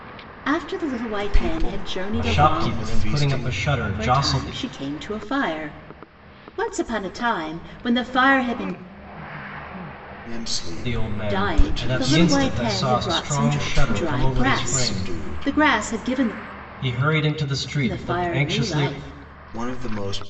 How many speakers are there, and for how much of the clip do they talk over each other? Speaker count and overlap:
3, about 44%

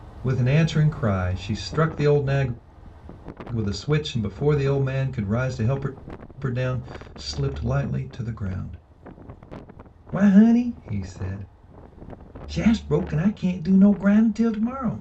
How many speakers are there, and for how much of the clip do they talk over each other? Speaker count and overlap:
1, no overlap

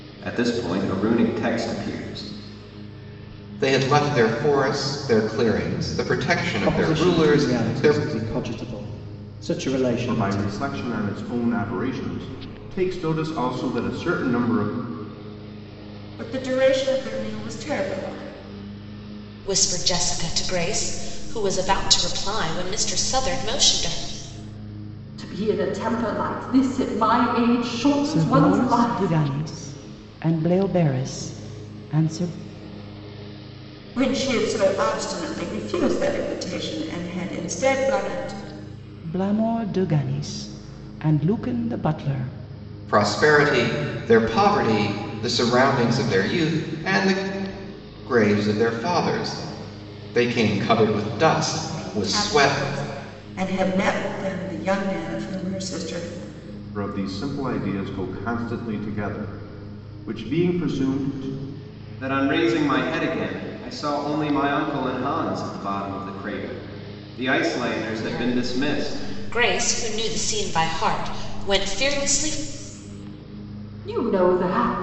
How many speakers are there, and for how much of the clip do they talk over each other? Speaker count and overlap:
8, about 7%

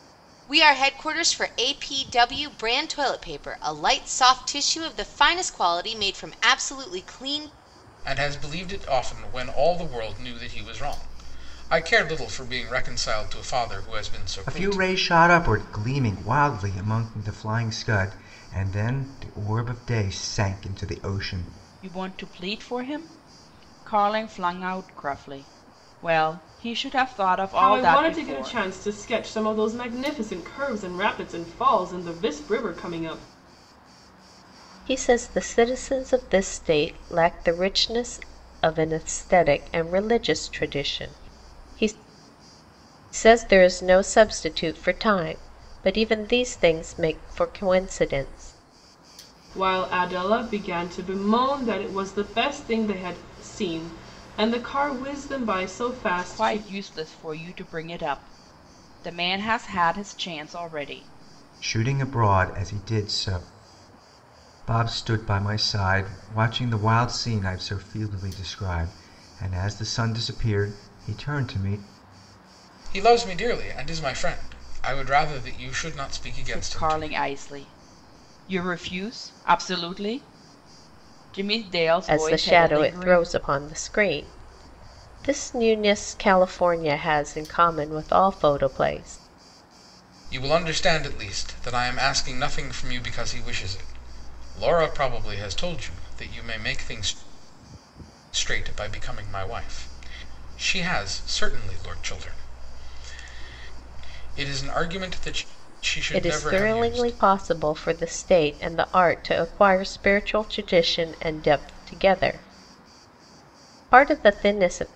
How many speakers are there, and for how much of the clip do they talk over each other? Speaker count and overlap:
6, about 5%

